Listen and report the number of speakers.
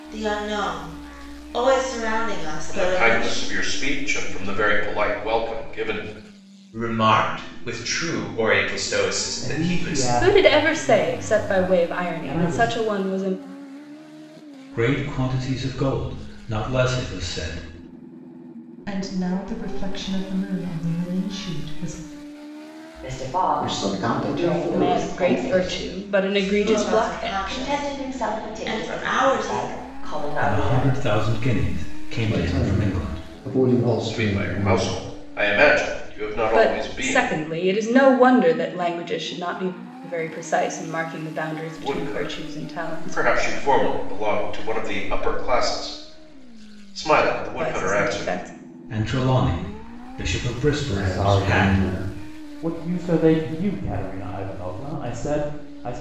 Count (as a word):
ten